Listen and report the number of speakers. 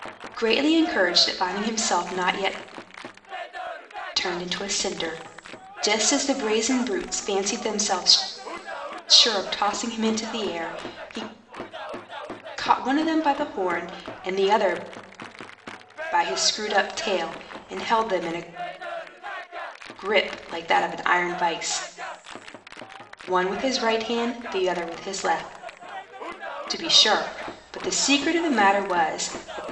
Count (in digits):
1